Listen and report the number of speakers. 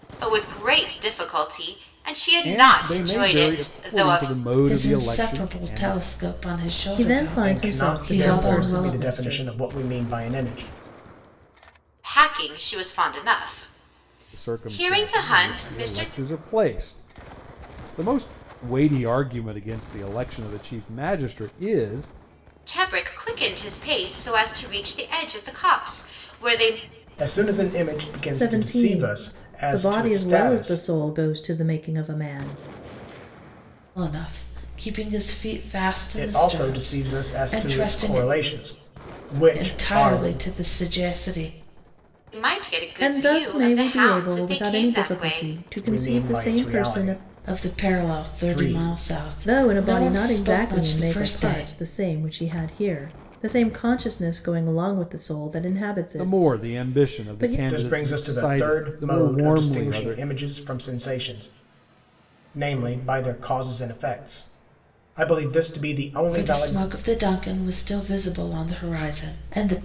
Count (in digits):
5